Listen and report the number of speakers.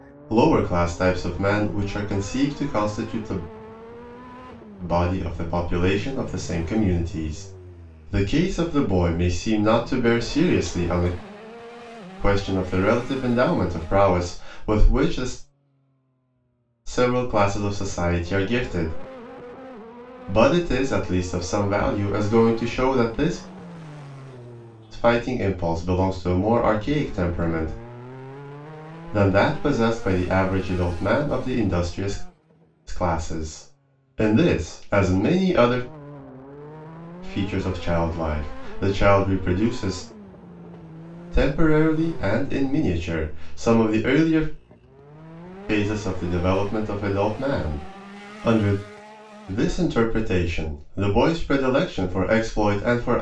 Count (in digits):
1